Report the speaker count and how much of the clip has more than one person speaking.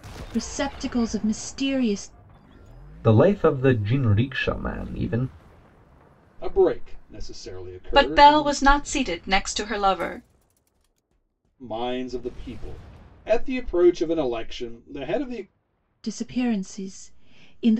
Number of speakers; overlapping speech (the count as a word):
four, about 4%